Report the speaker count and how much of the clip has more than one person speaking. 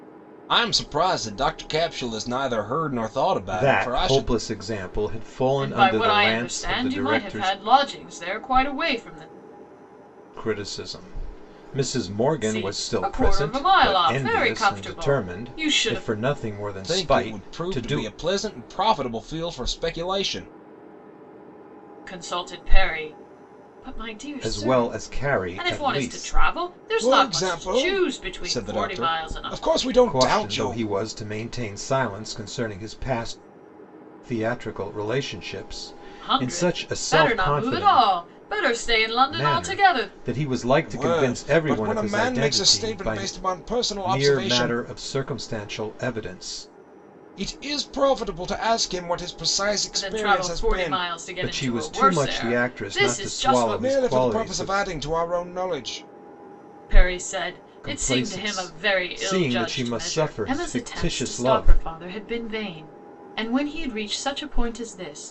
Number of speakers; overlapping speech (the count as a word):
three, about 42%